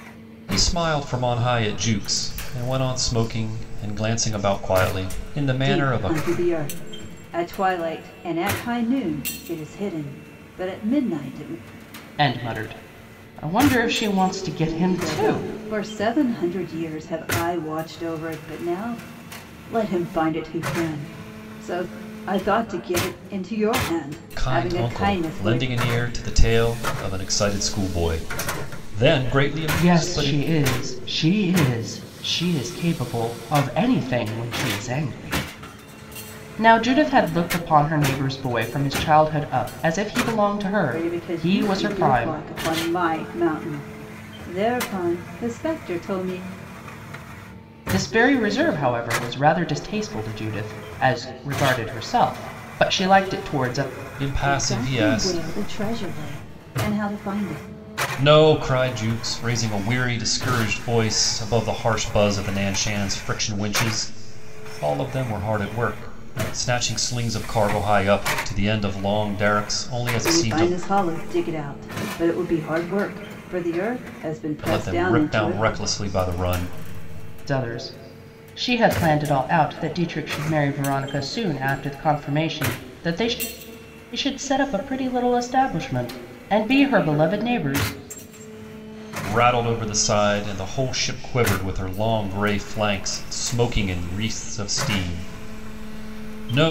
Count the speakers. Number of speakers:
three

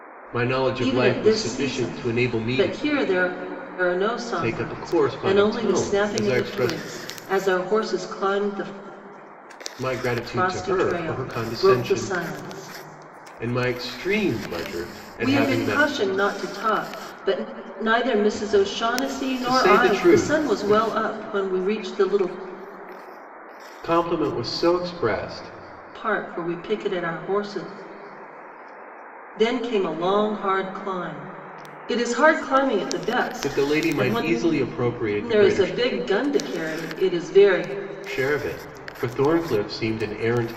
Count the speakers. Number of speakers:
two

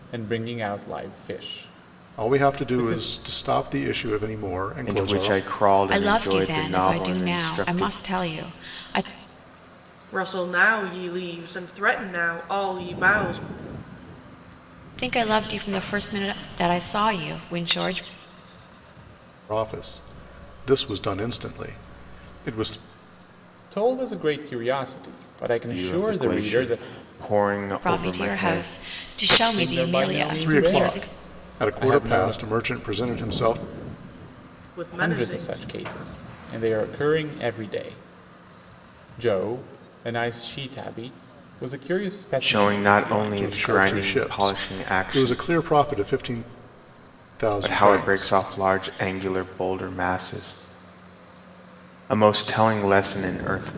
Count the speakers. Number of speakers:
five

